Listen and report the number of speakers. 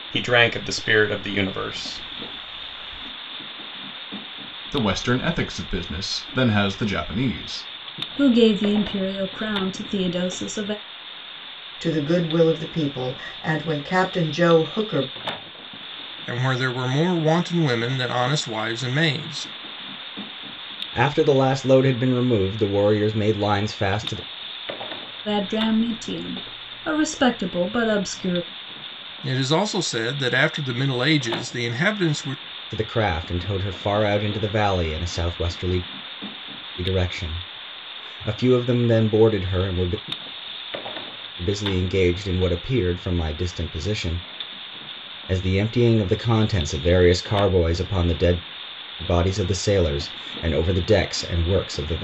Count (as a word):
six